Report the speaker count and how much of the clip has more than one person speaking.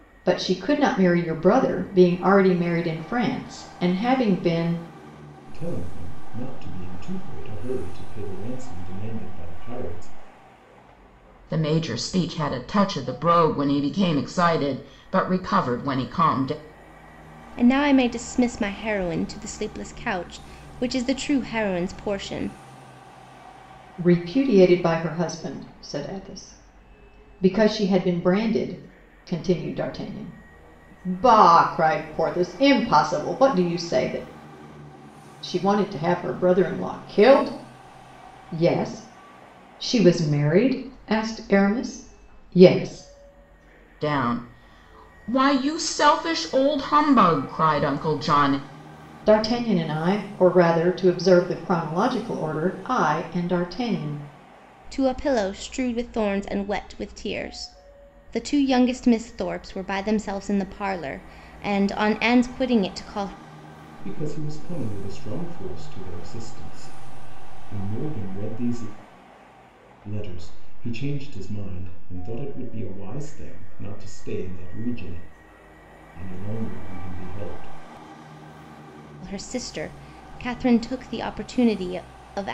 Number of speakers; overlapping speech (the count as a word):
four, no overlap